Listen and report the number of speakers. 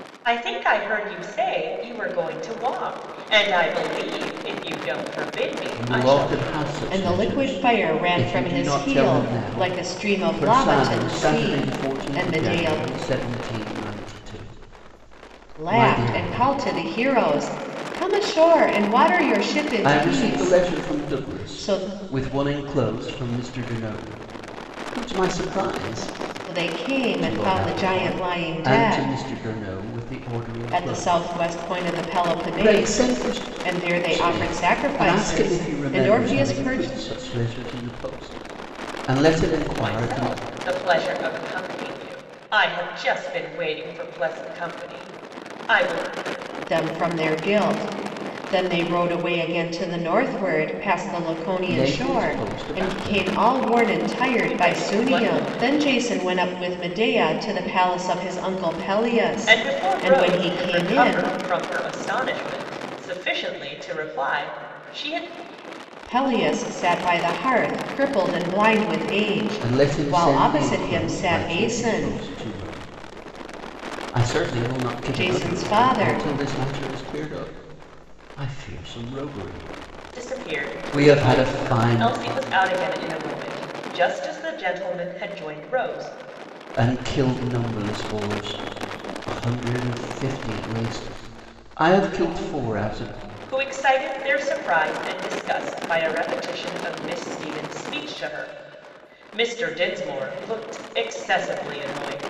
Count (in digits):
3